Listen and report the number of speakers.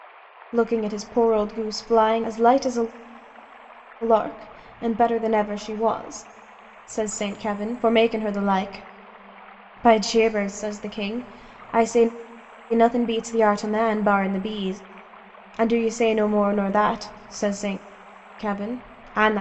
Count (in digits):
1